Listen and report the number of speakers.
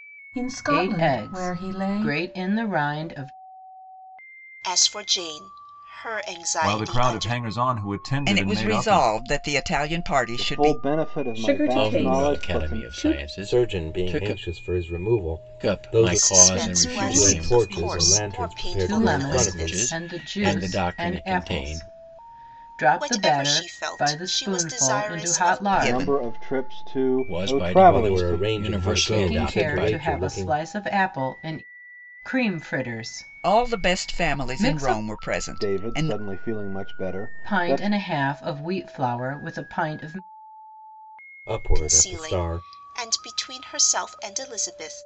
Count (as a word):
nine